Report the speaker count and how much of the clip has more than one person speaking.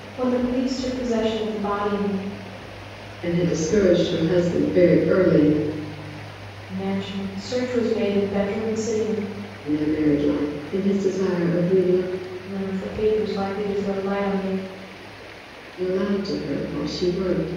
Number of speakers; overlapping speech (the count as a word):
two, no overlap